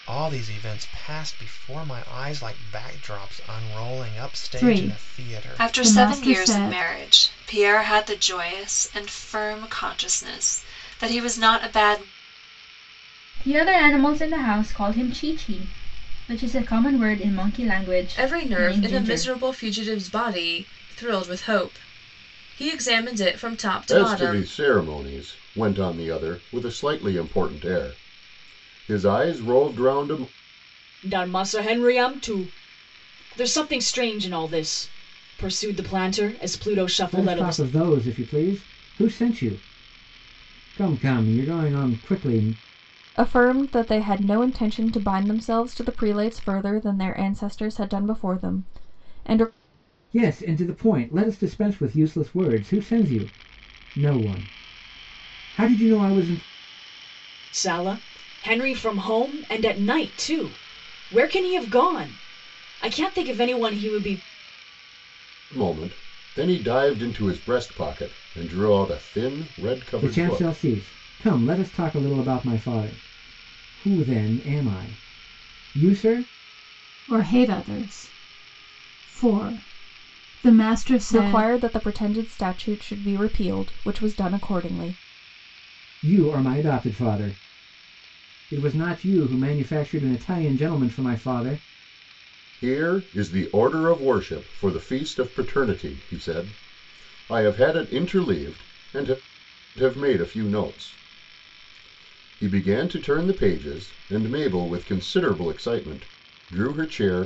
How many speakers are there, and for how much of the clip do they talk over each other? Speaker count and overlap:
9, about 5%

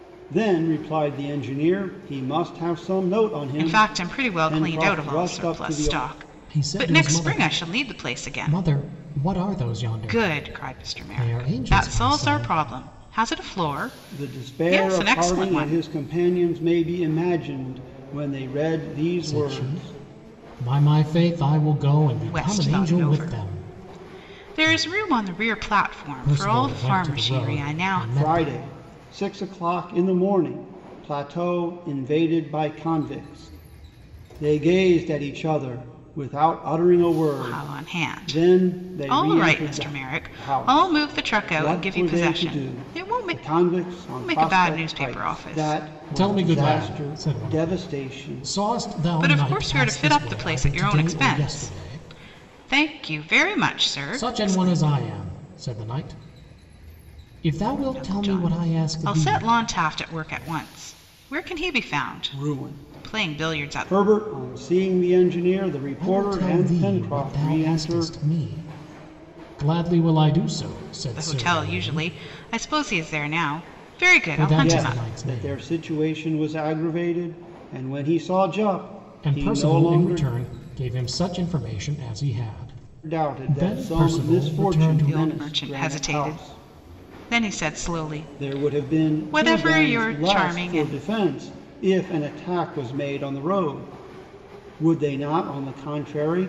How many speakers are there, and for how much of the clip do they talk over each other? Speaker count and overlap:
3, about 44%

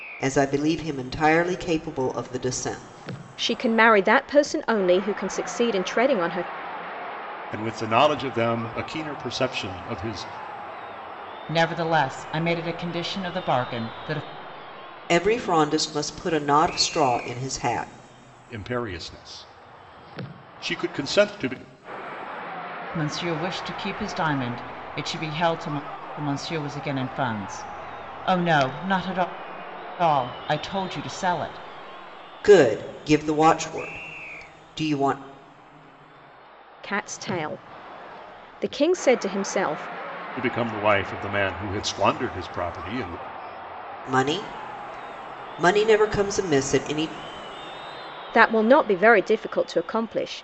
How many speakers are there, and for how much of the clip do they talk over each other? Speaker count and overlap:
4, no overlap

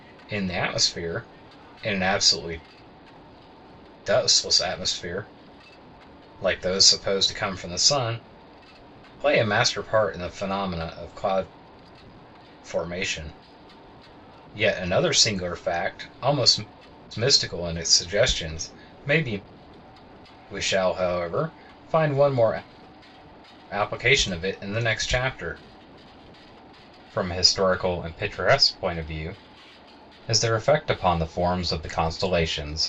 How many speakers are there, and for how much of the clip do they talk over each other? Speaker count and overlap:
1, no overlap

